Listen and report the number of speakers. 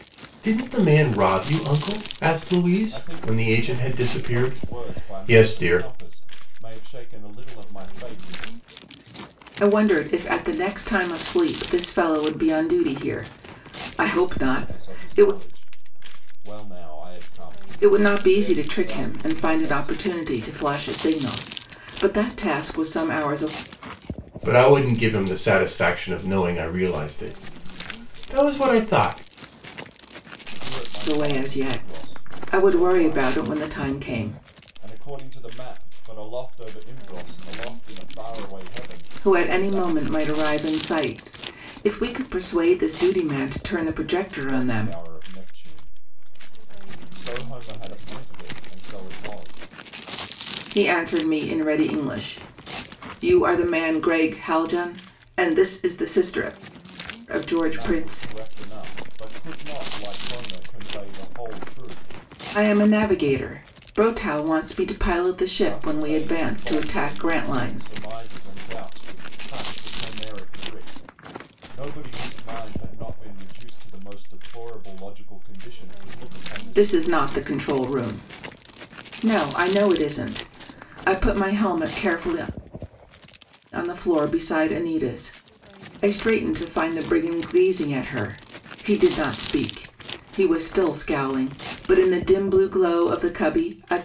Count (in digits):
3